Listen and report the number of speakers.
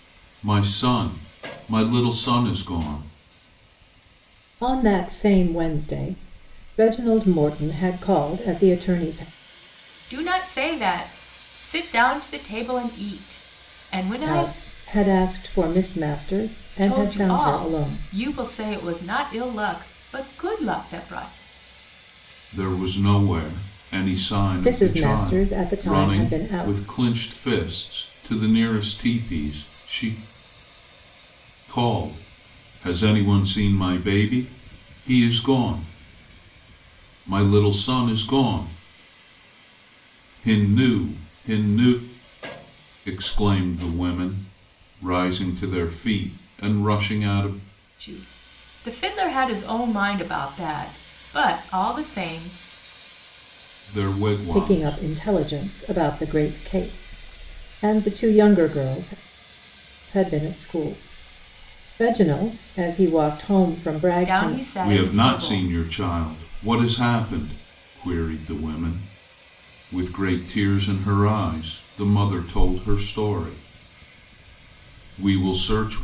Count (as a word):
three